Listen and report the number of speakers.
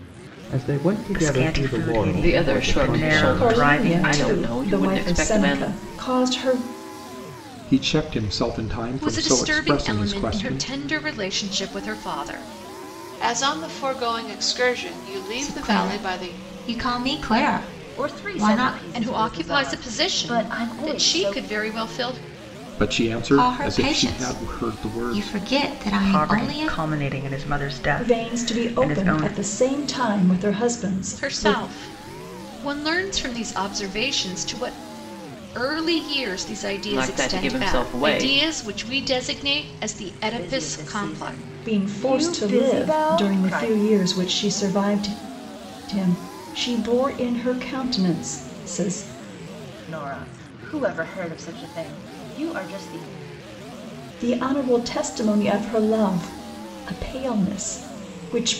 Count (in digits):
9